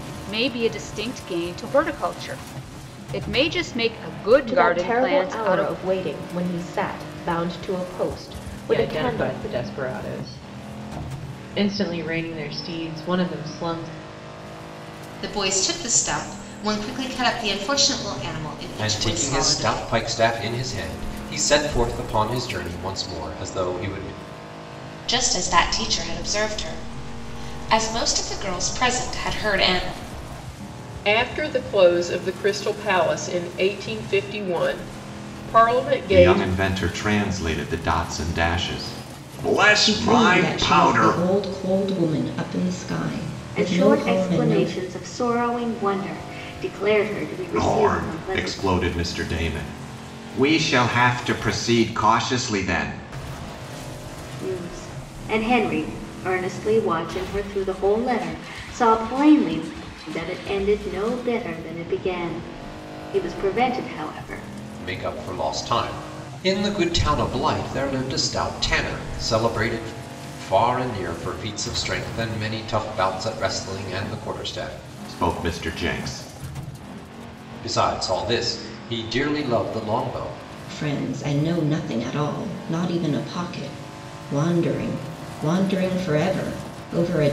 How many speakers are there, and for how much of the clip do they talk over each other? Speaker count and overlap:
ten, about 9%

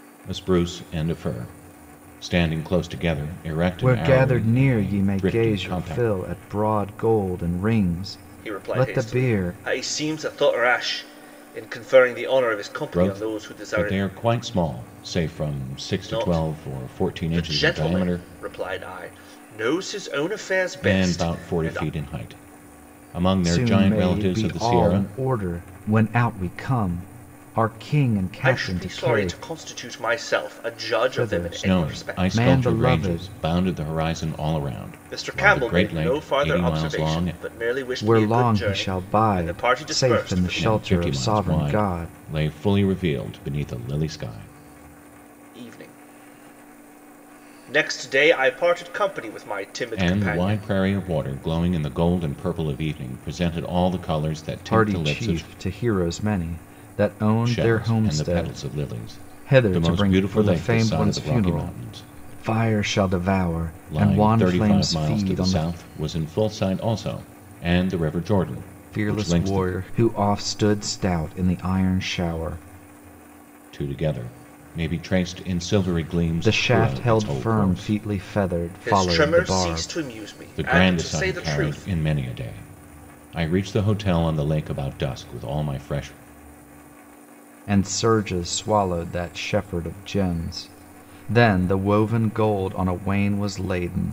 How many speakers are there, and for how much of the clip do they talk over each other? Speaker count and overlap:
three, about 35%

